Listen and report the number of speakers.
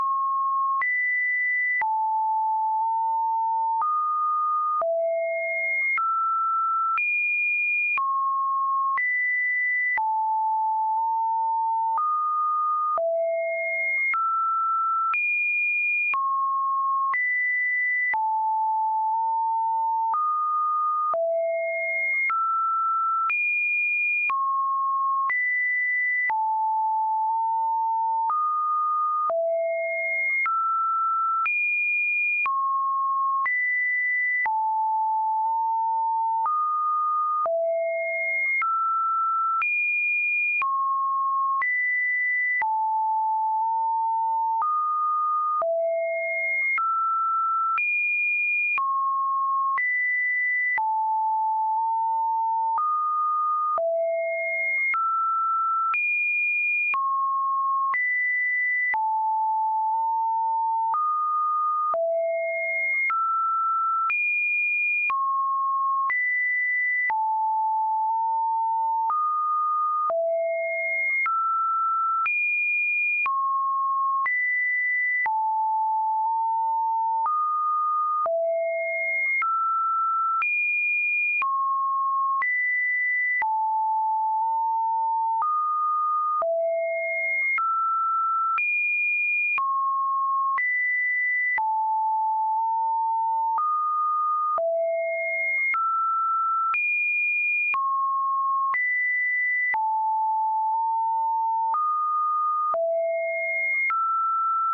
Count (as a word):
zero